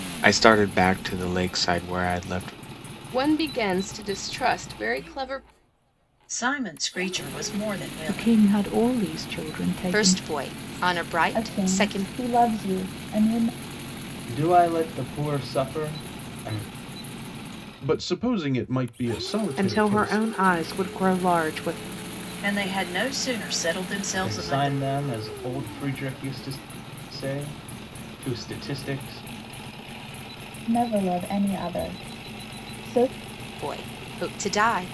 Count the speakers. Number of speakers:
9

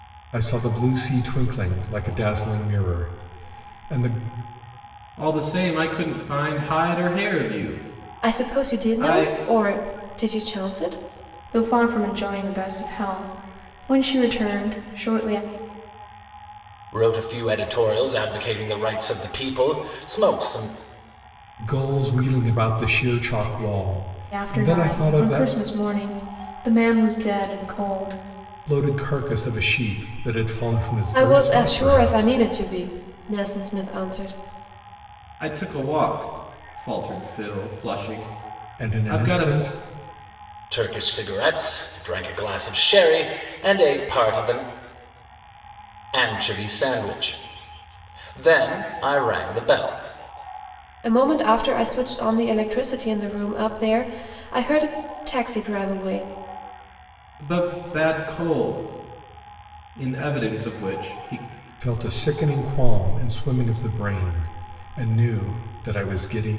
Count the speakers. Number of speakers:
5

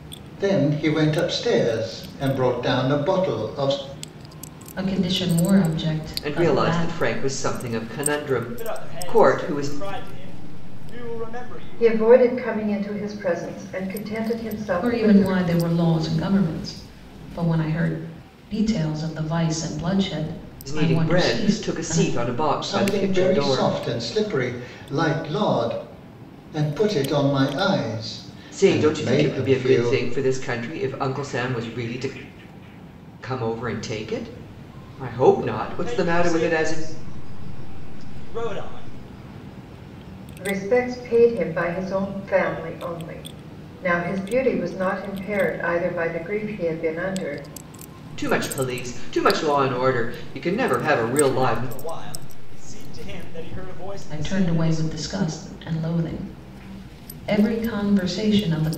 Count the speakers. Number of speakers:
5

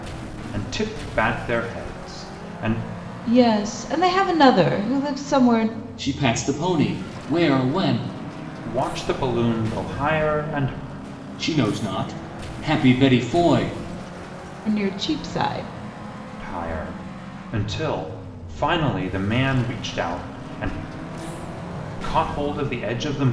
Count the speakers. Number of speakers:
3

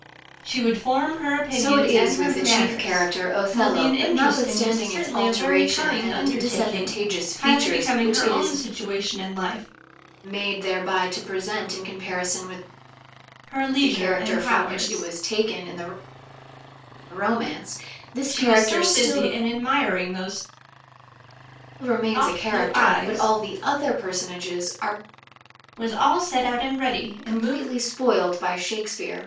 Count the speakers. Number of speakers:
2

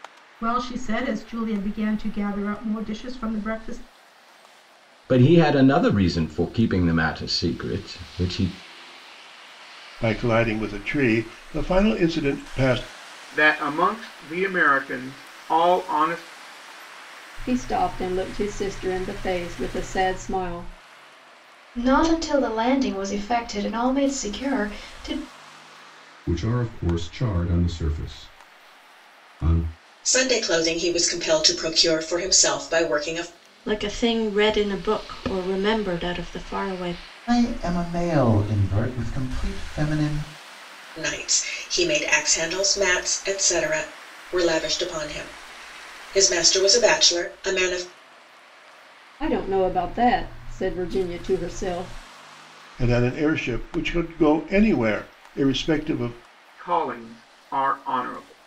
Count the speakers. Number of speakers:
10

